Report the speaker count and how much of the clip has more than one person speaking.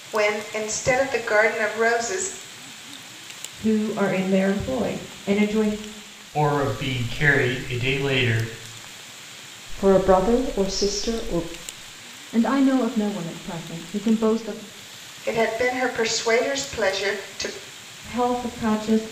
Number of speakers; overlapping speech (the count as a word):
five, no overlap